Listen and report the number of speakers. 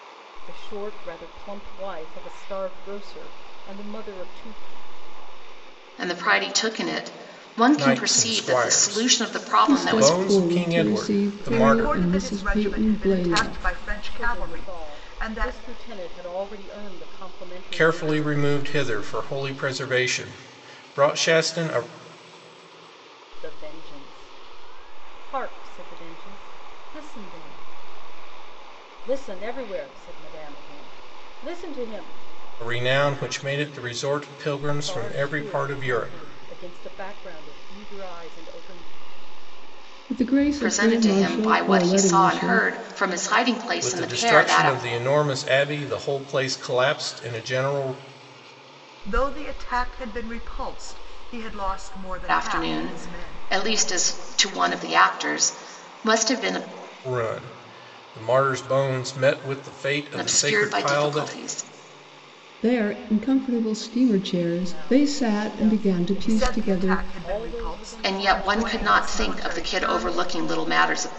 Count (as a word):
five